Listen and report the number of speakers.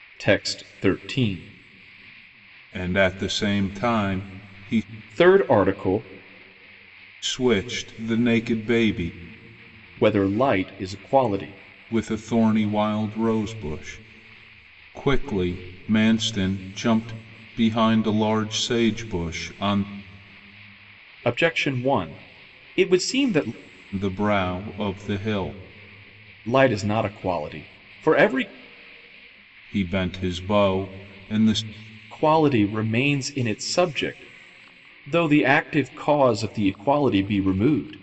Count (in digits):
2